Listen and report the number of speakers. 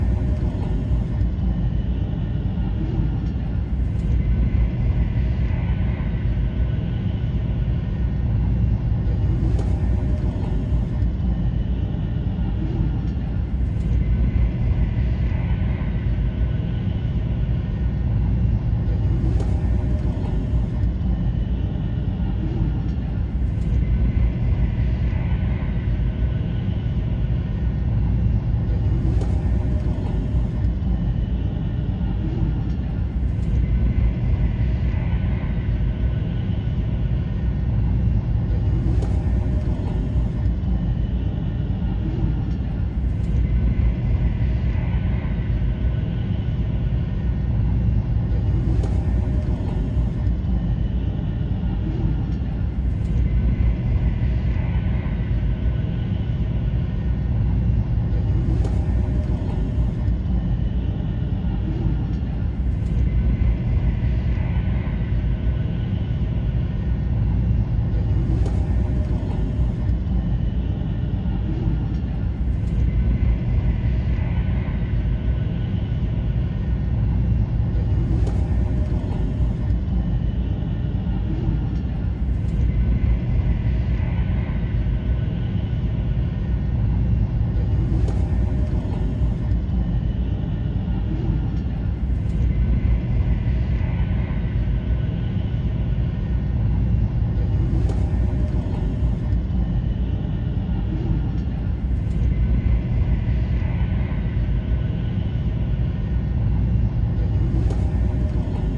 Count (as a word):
zero